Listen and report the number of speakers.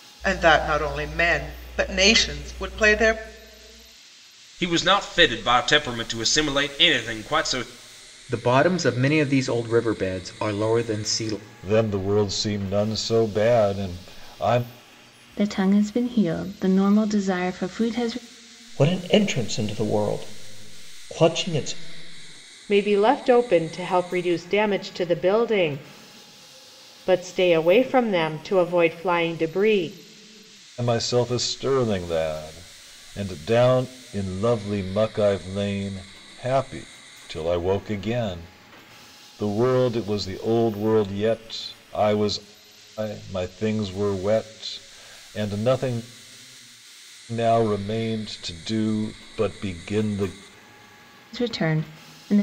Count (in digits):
7